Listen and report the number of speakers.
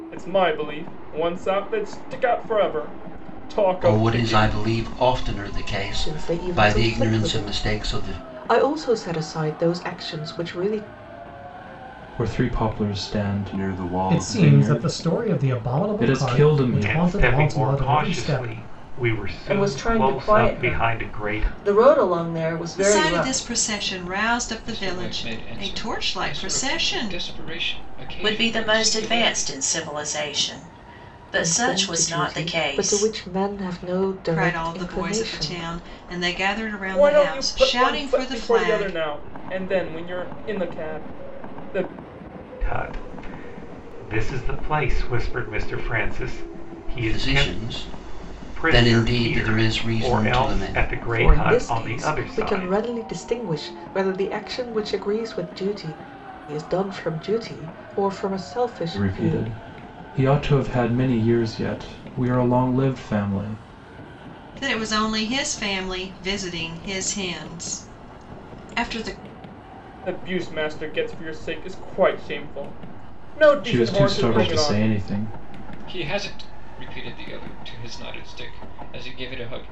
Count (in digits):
10